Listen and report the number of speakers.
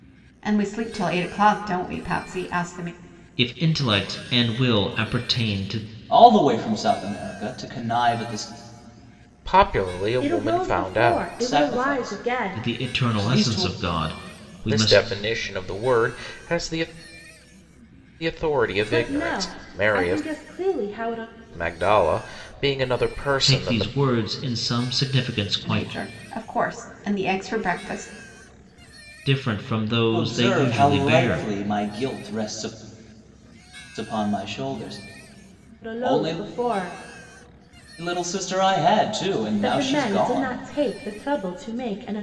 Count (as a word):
five